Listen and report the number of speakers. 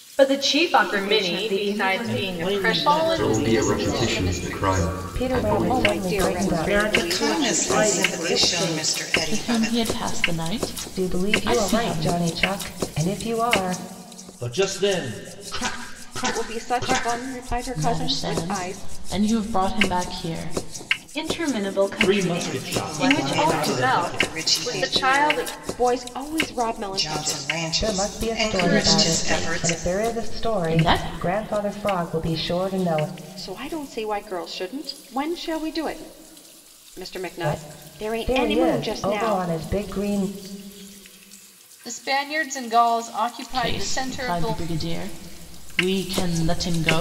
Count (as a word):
ten